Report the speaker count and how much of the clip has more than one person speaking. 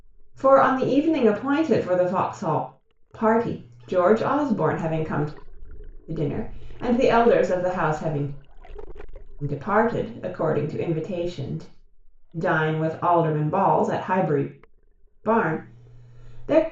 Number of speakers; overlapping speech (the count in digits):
1, no overlap